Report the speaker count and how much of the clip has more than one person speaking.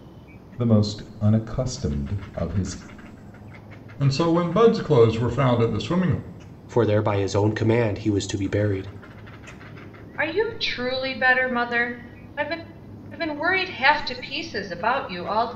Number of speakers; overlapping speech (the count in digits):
4, no overlap